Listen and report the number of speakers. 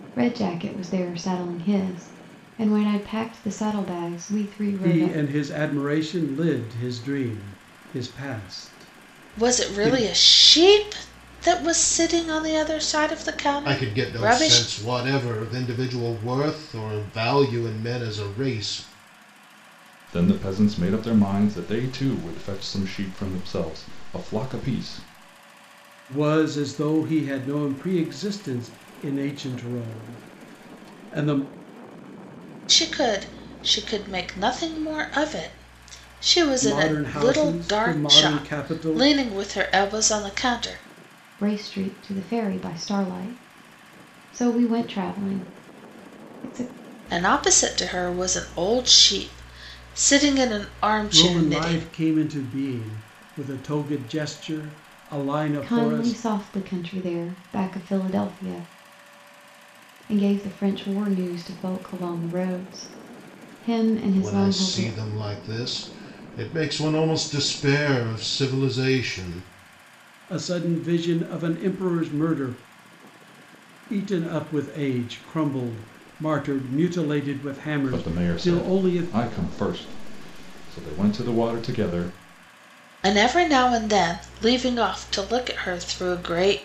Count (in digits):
5